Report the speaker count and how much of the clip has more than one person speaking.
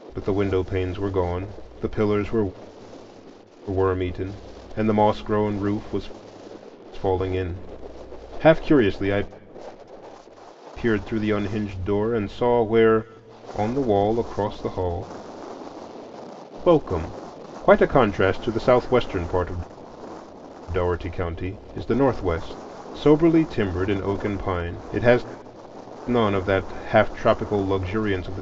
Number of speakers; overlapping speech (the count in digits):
1, no overlap